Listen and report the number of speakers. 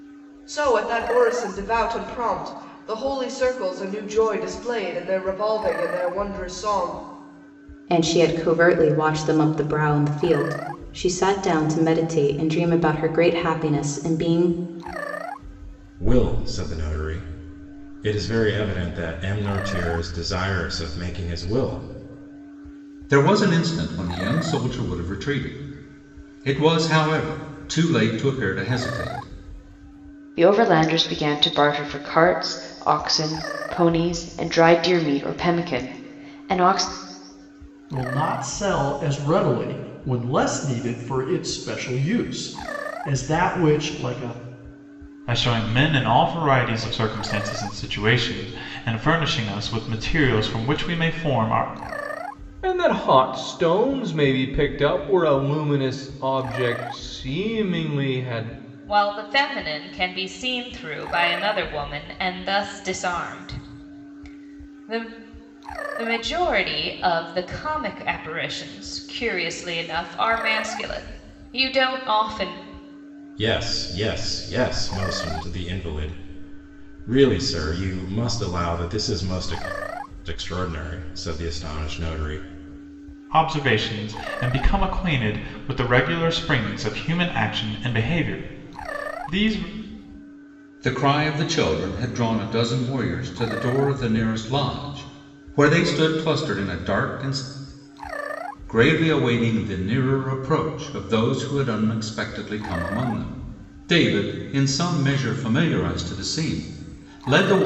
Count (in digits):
9